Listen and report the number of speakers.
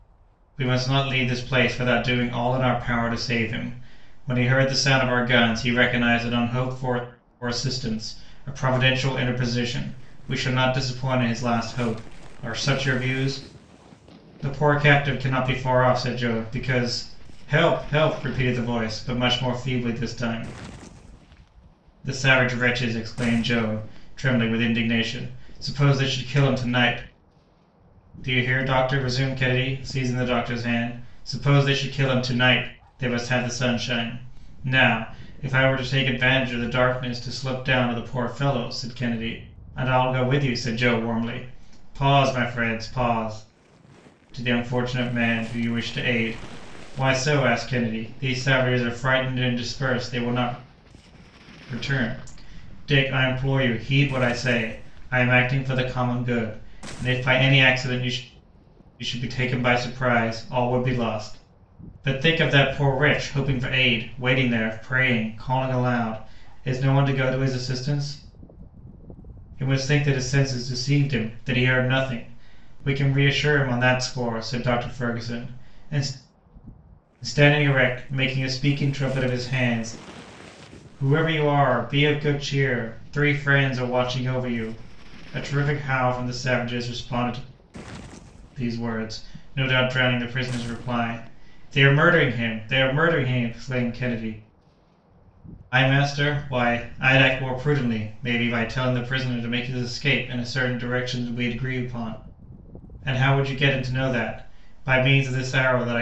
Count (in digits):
1